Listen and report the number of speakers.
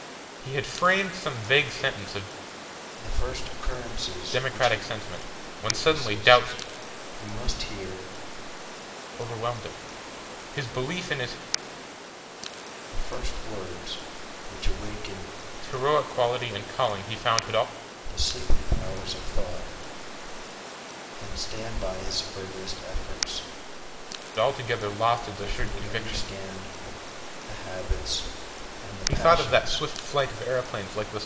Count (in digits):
2